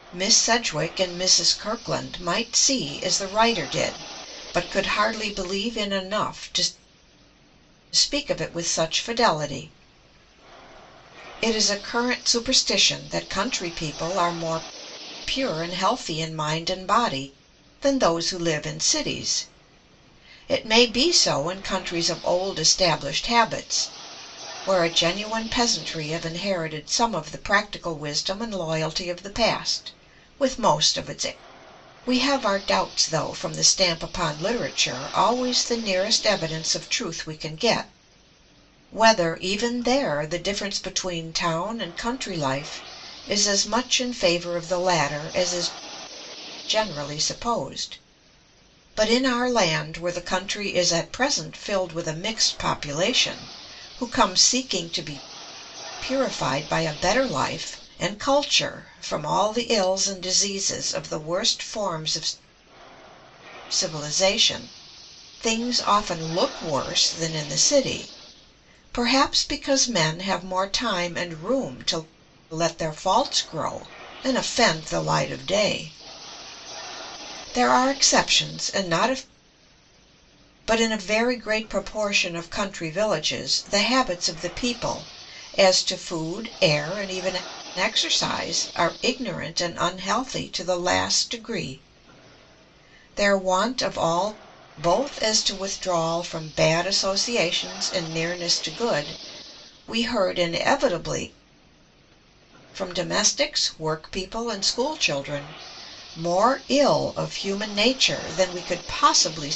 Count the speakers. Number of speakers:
1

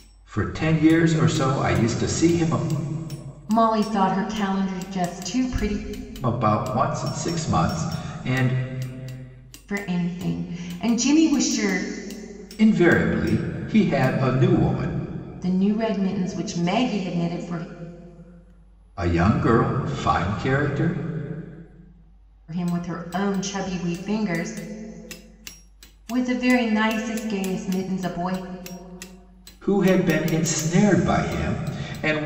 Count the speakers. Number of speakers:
2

